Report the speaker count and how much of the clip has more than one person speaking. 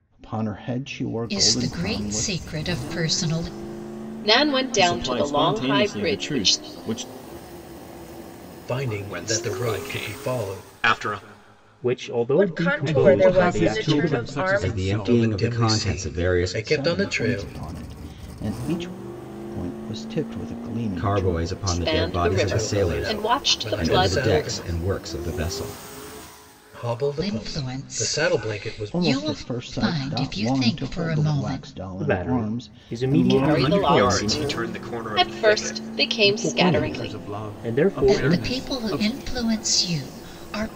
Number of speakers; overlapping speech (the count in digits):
10, about 60%